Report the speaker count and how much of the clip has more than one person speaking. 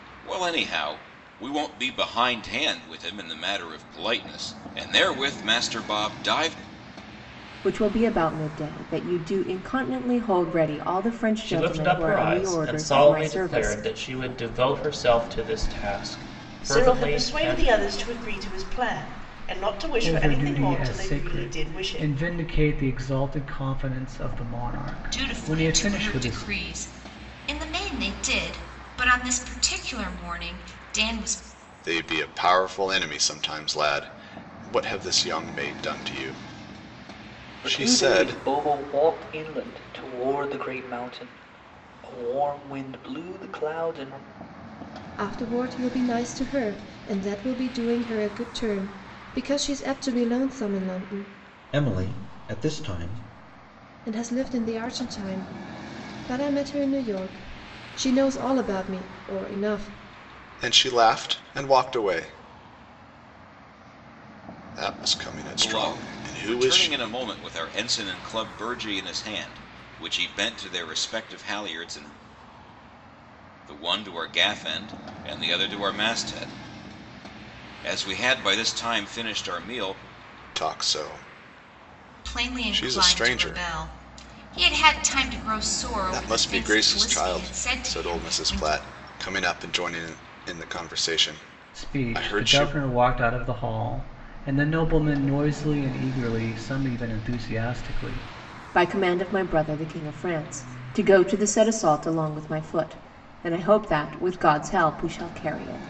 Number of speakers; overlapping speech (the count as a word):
ten, about 14%